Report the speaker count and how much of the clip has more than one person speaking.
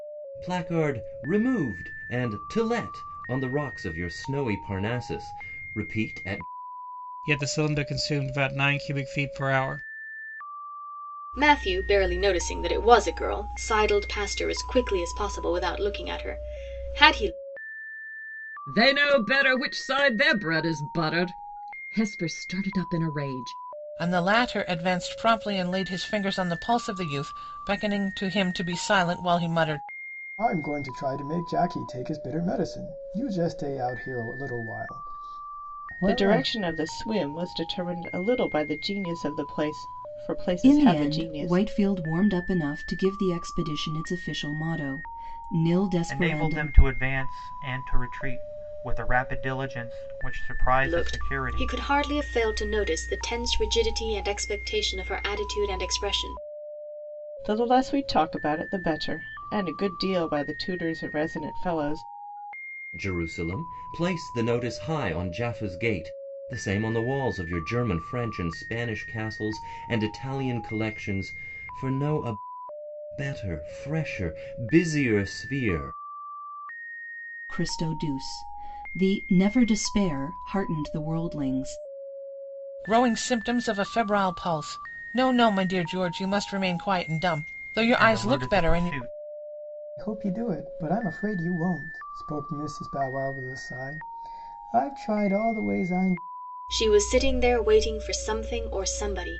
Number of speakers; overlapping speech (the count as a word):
nine, about 4%